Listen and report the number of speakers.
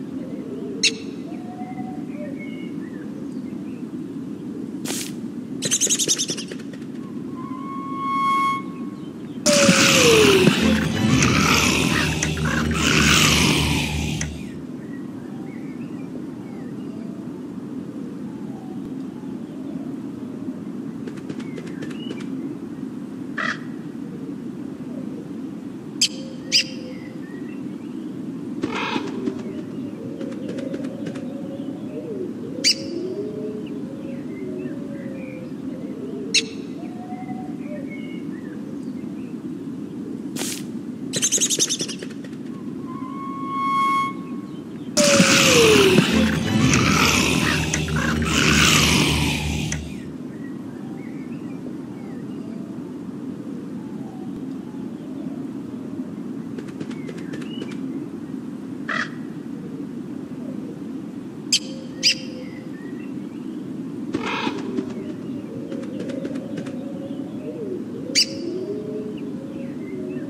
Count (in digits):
0